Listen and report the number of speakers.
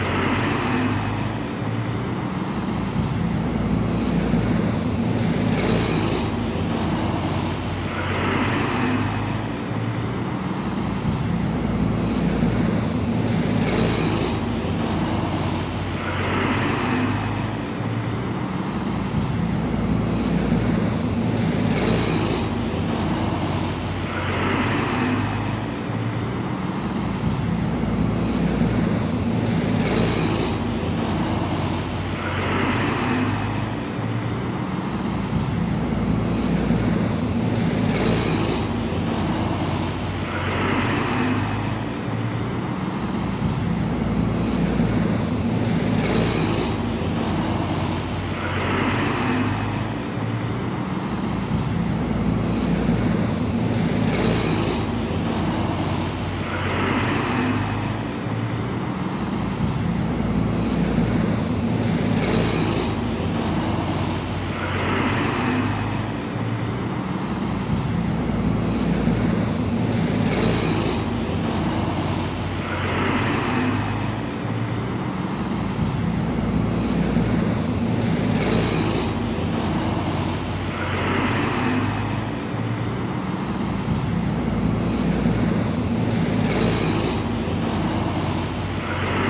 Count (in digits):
0